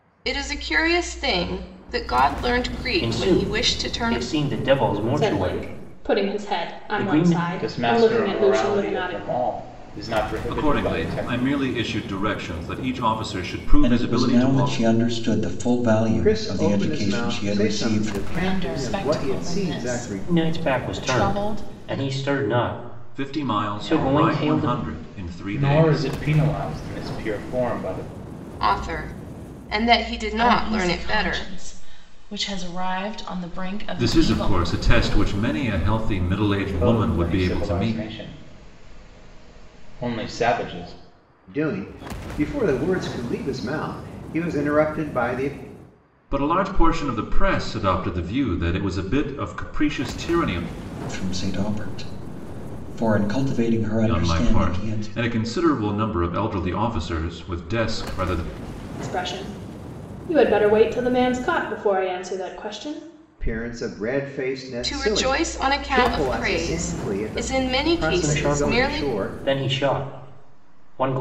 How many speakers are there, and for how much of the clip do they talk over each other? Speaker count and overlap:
8, about 35%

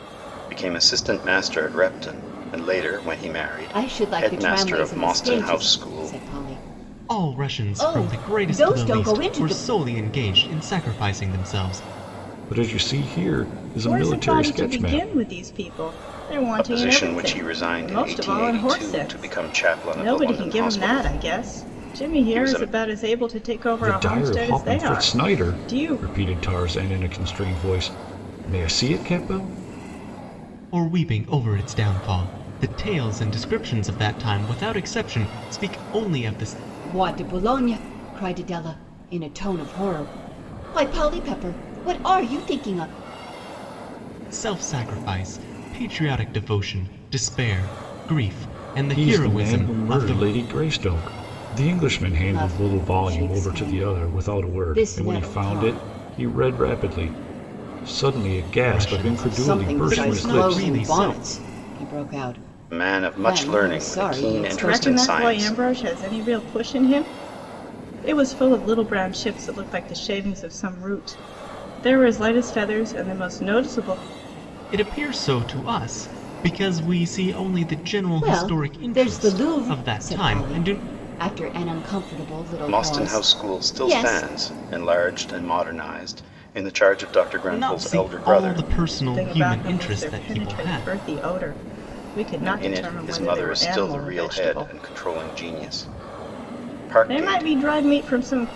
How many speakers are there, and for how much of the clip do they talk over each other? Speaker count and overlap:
5, about 35%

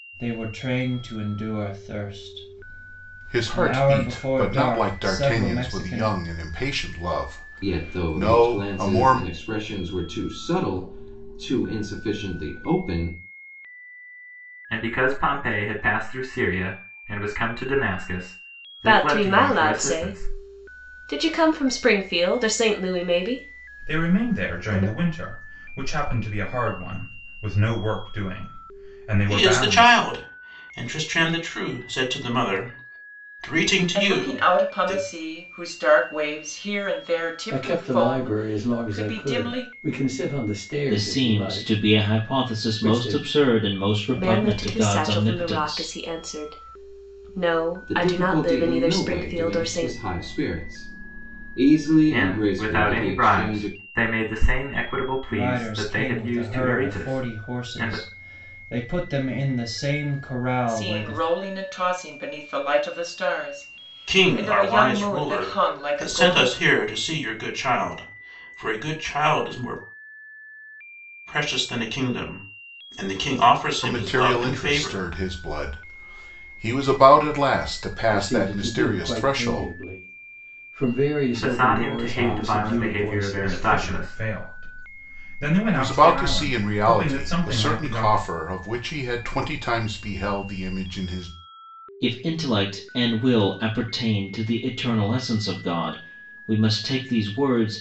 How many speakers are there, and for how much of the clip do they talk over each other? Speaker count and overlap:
10, about 34%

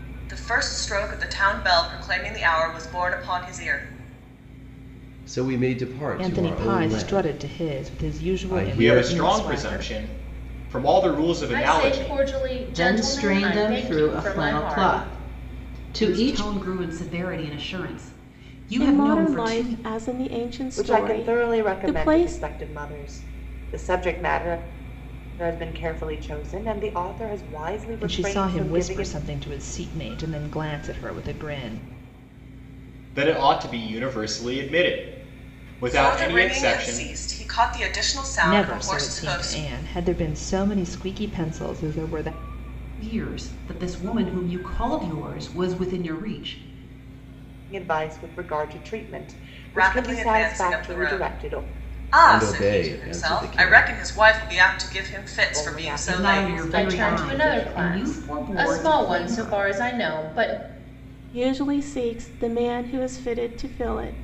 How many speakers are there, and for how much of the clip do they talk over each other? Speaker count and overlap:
9, about 33%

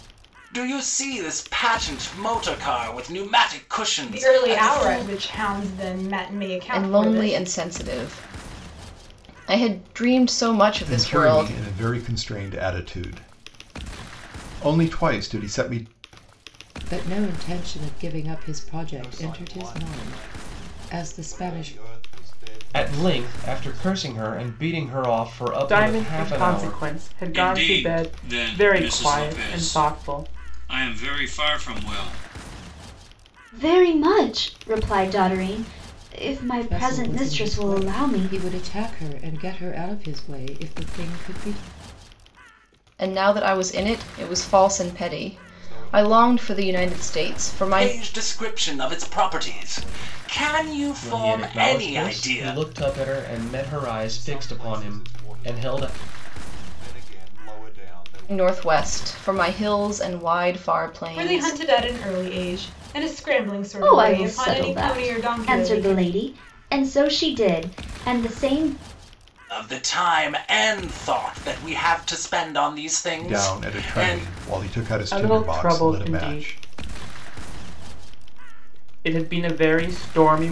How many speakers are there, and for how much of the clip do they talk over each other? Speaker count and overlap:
10, about 33%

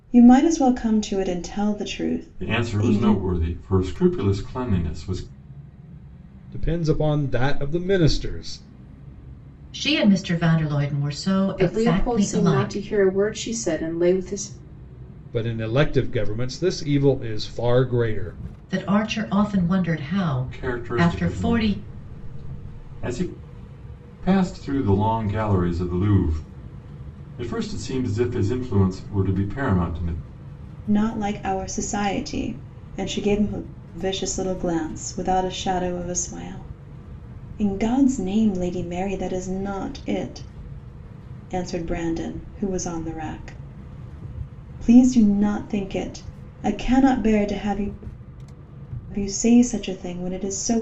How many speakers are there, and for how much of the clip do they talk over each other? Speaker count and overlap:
5, about 7%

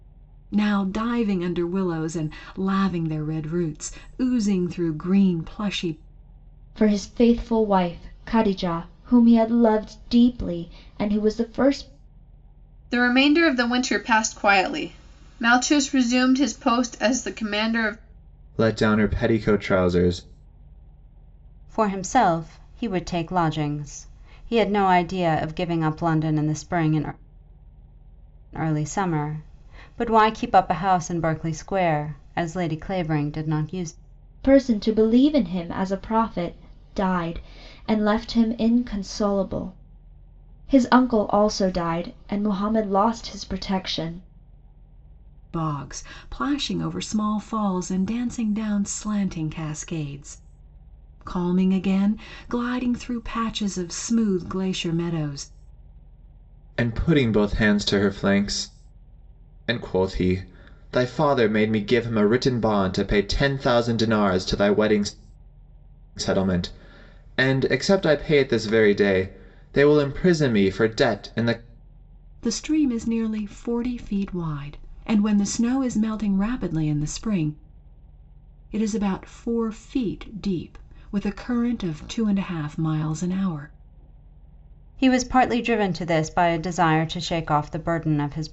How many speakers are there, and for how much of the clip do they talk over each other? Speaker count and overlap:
5, no overlap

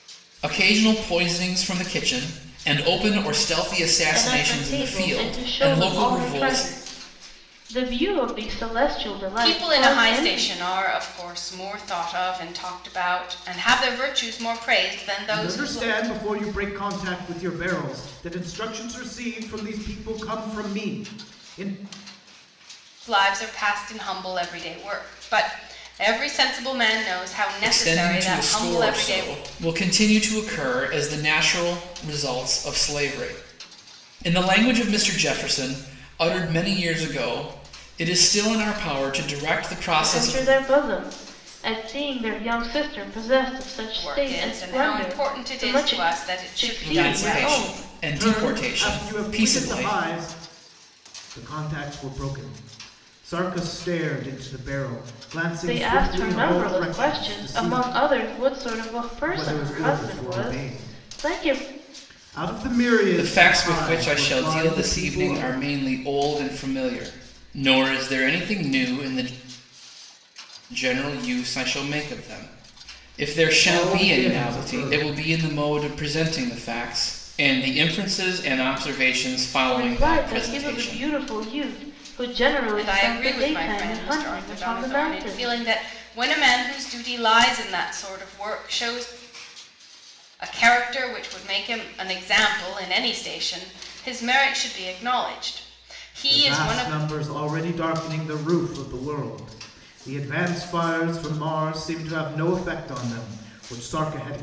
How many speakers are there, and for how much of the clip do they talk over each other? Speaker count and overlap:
4, about 24%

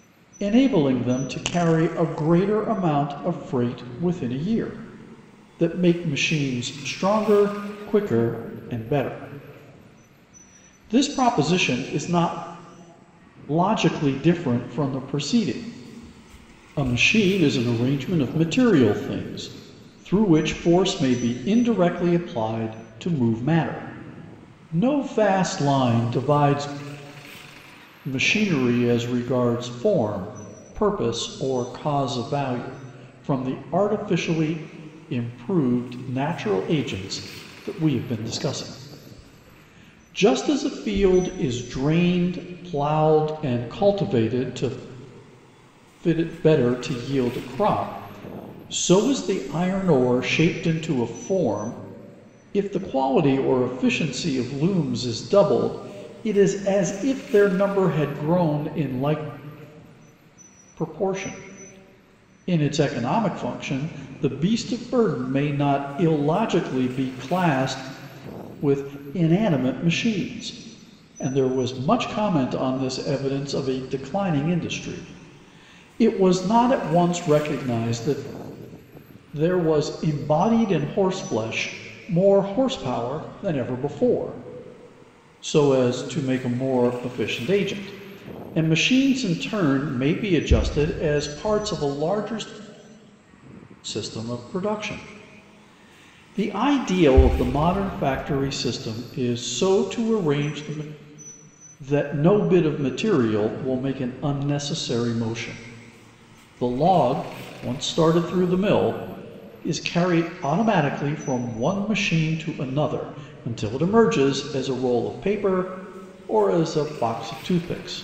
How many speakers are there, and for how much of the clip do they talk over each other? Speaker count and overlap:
1, no overlap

